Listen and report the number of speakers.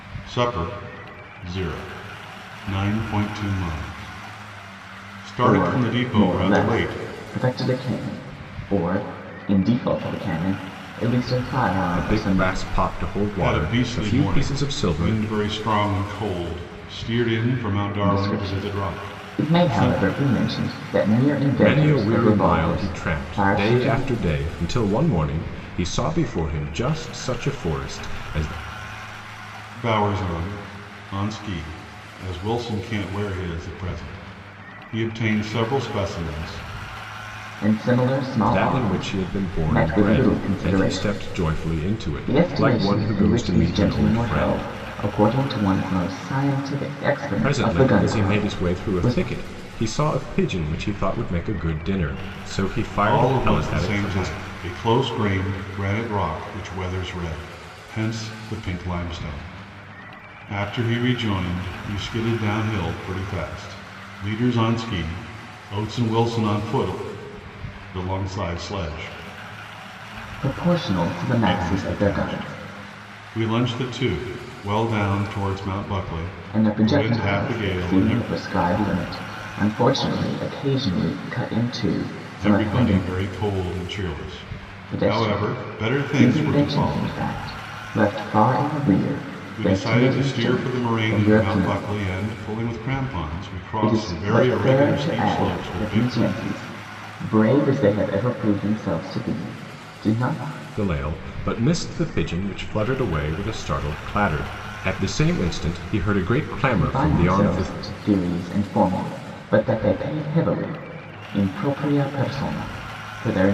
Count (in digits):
3